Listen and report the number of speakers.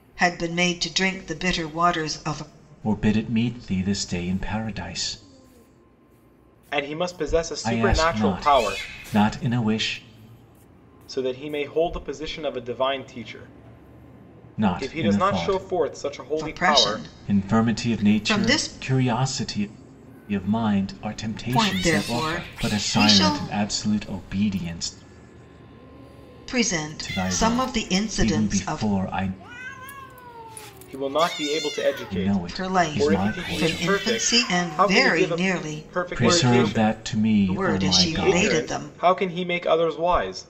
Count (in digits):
3